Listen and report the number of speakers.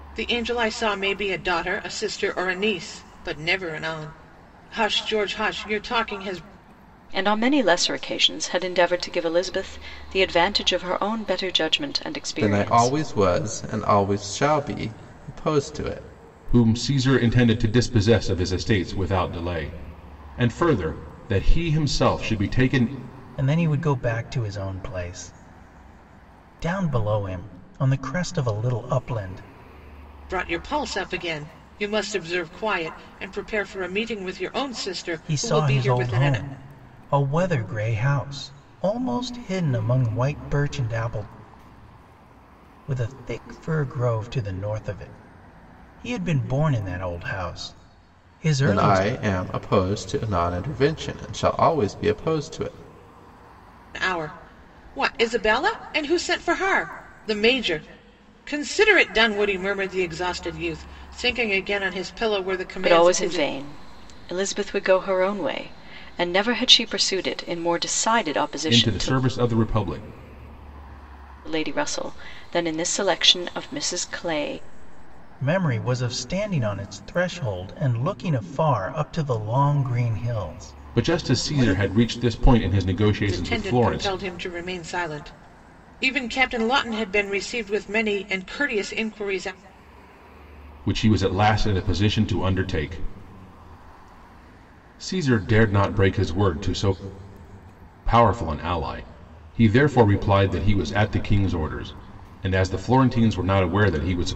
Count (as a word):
five